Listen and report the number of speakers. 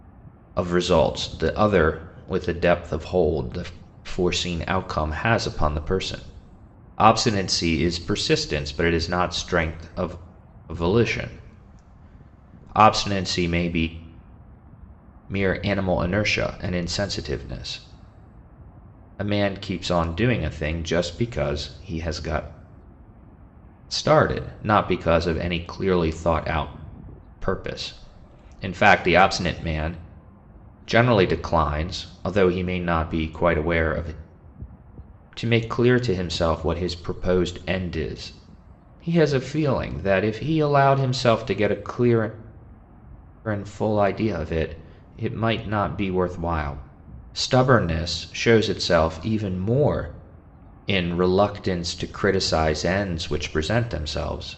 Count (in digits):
1